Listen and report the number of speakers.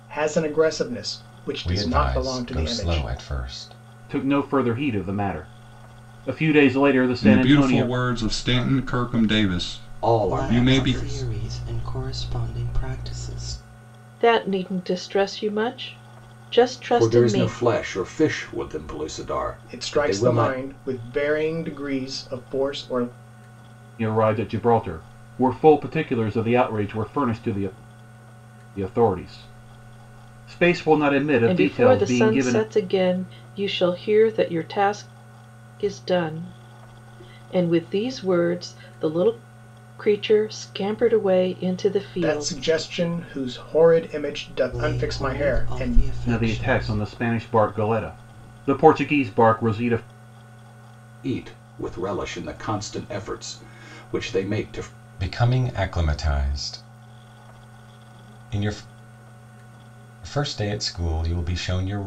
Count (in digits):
7